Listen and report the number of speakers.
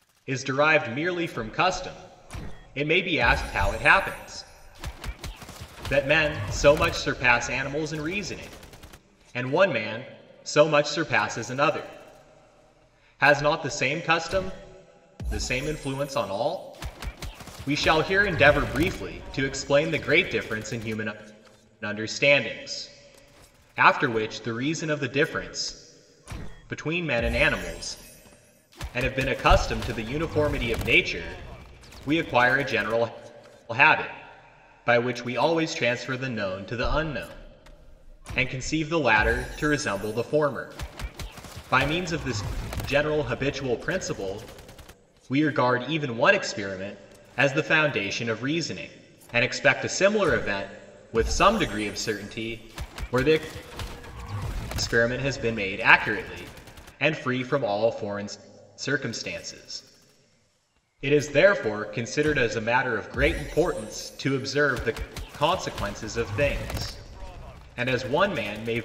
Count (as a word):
one